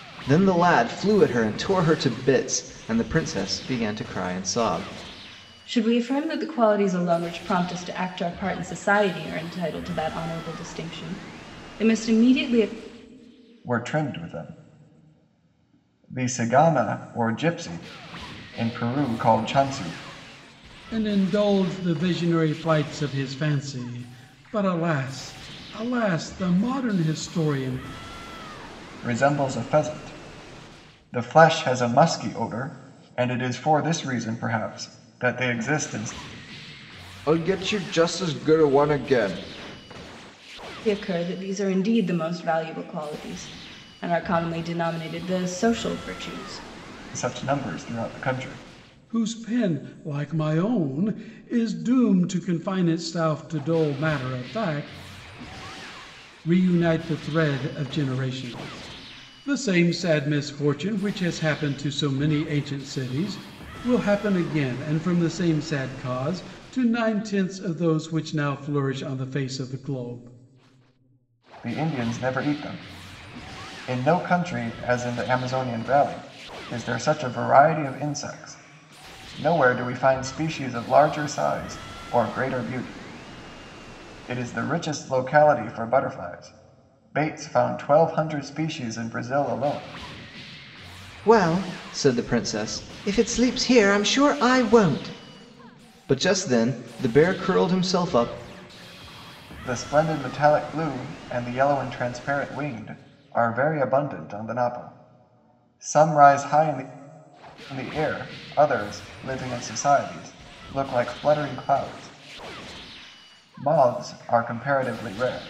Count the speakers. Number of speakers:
4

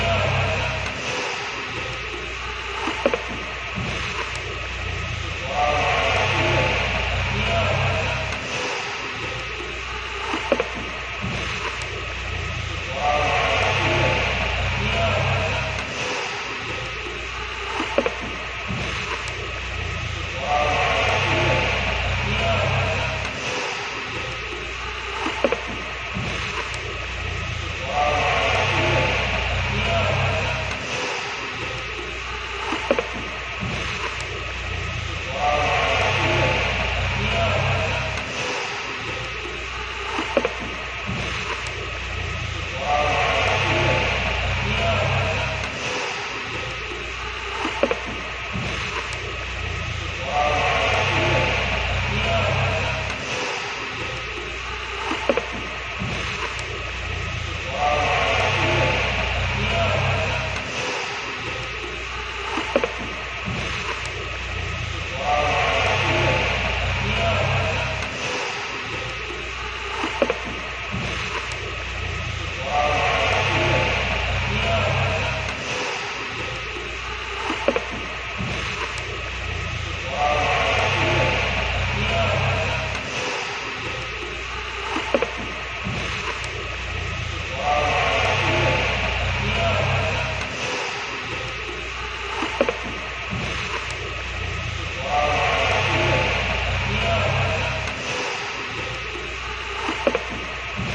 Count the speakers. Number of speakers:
0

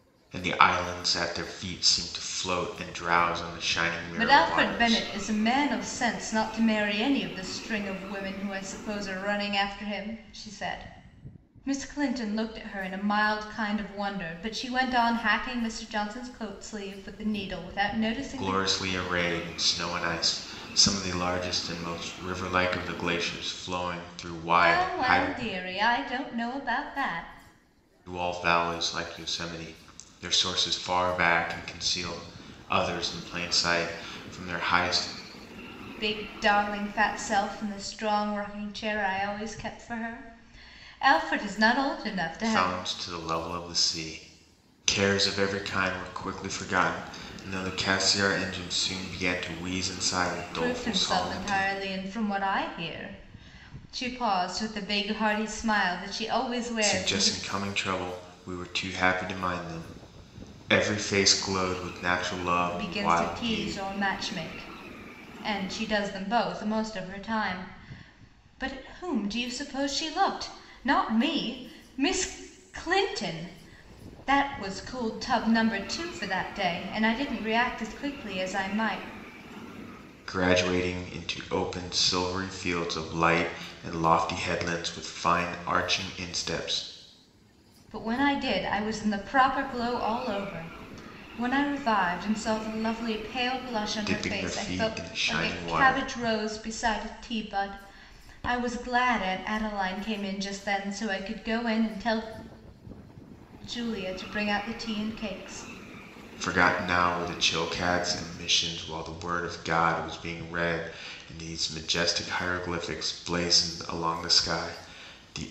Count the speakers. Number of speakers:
2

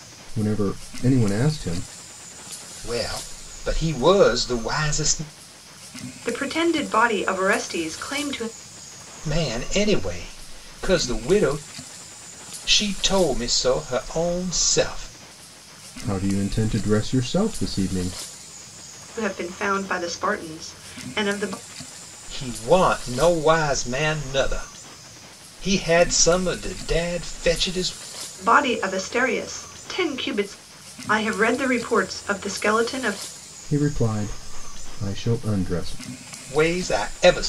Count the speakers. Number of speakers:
3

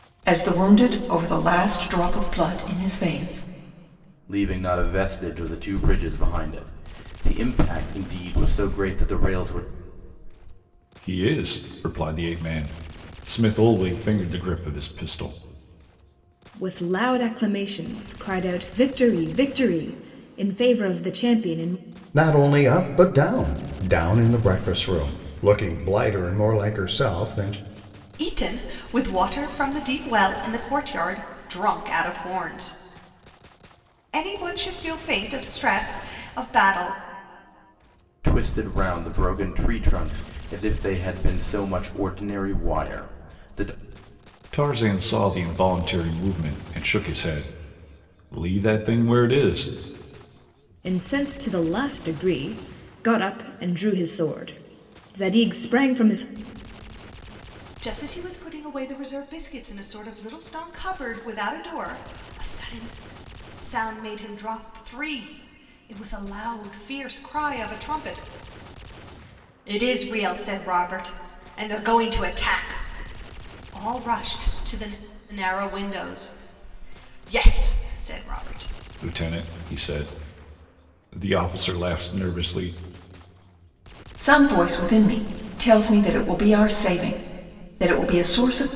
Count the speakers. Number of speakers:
6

